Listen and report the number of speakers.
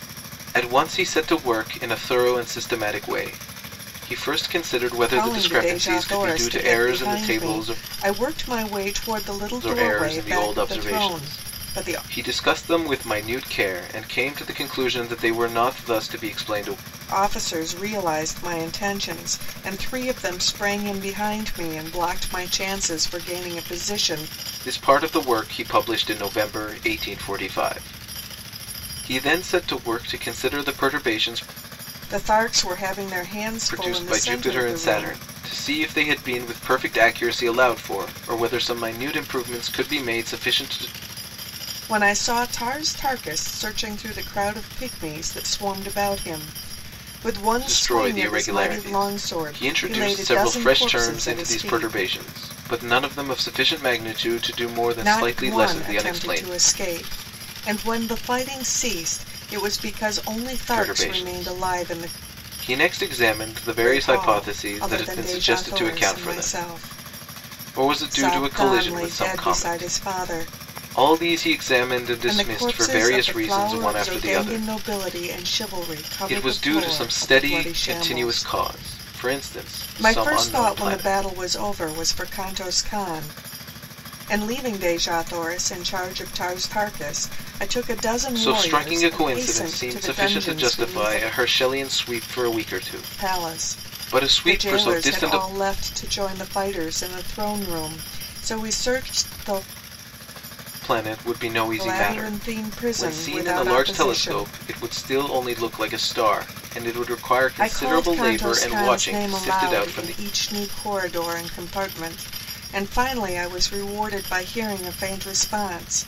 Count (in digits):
2